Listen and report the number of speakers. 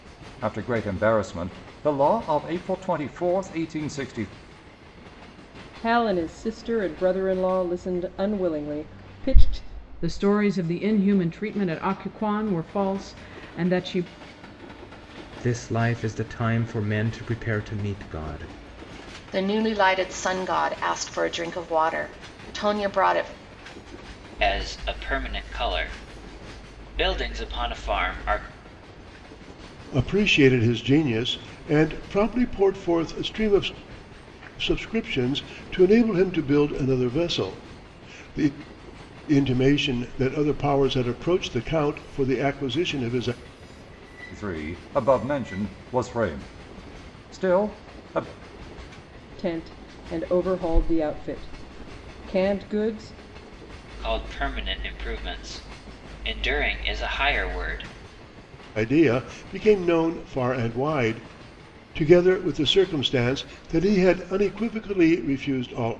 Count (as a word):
seven